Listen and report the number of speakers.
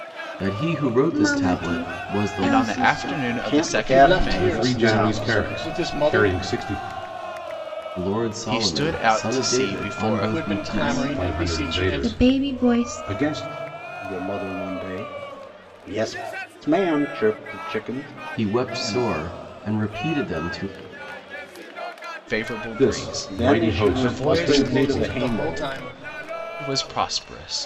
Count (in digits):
6